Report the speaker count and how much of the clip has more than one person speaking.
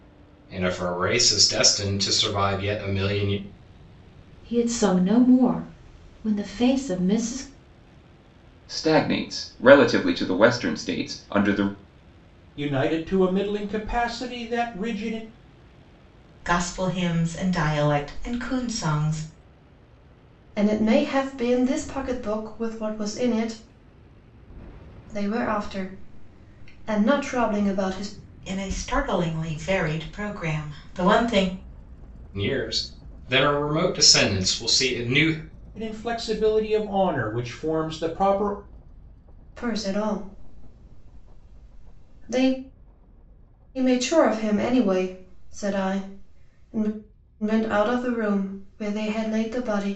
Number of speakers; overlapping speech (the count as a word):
six, no overlap